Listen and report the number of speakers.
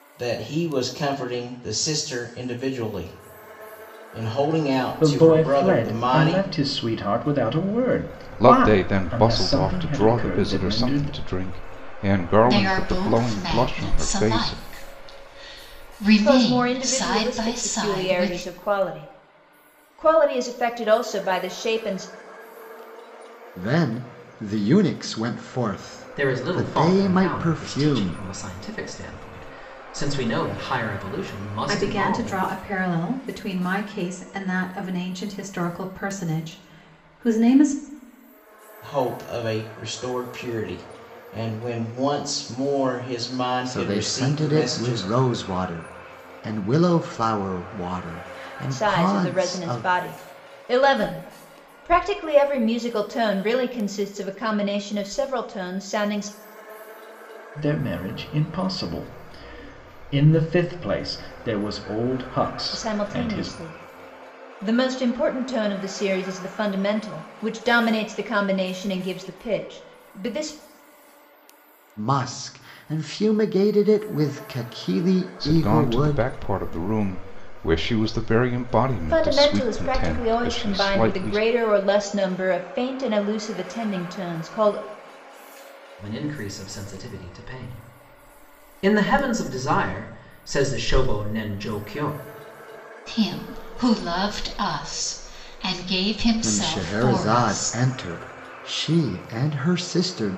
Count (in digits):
8